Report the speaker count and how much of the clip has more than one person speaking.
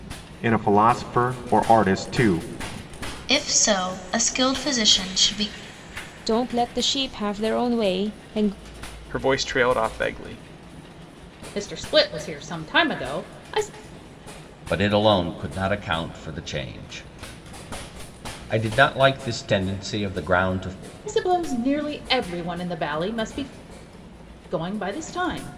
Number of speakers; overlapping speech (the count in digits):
6, no overlap